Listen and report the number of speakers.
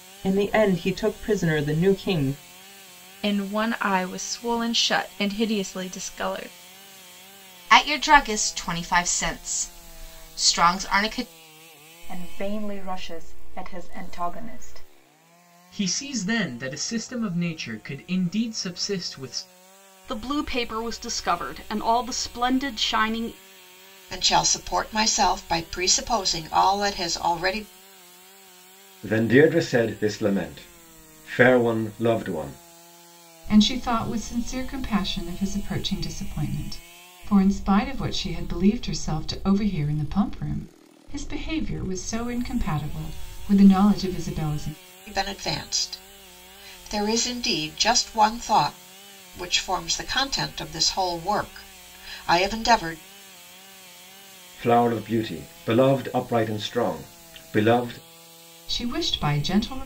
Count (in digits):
9